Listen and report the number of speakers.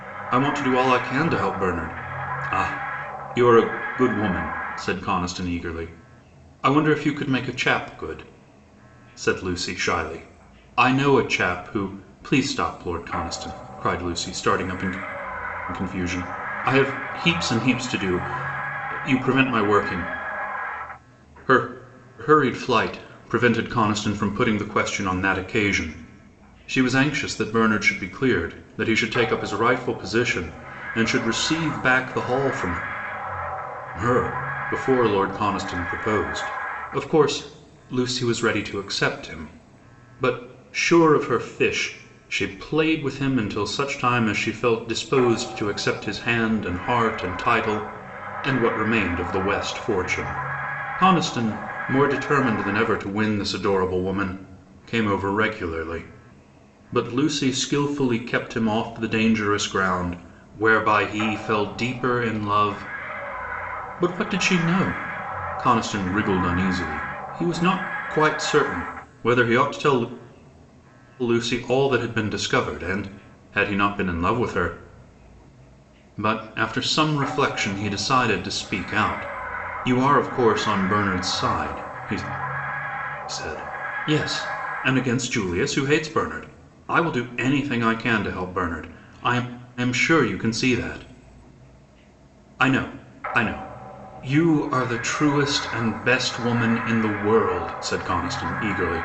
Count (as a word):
one